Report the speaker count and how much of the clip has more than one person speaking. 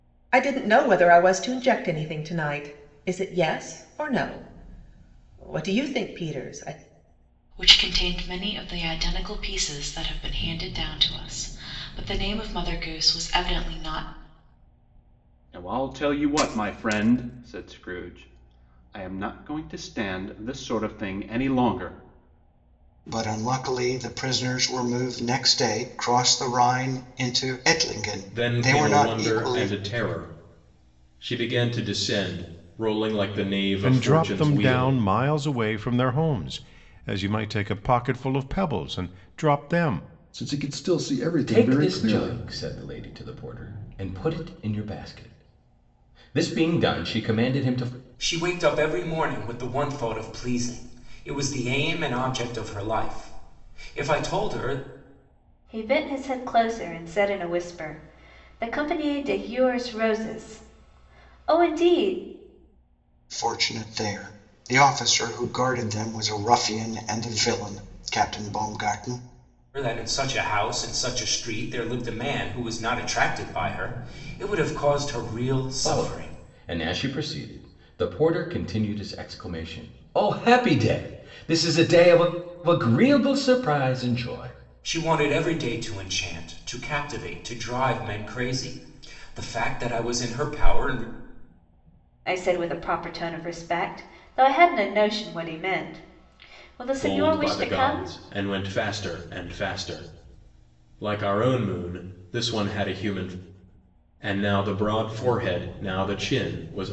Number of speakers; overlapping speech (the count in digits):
10, about 5%